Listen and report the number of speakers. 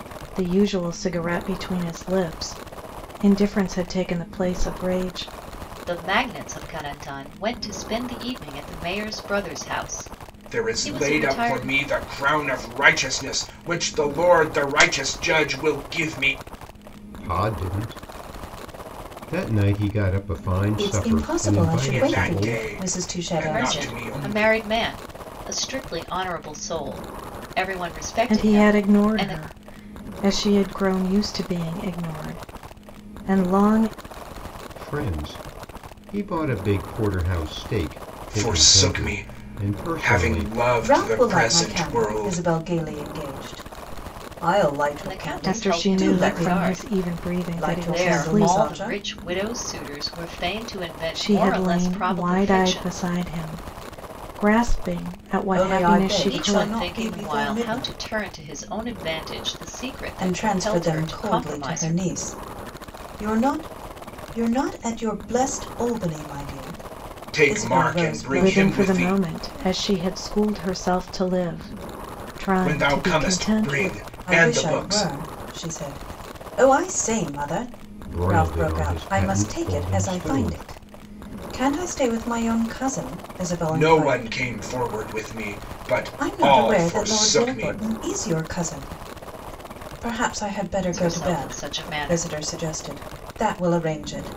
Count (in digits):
5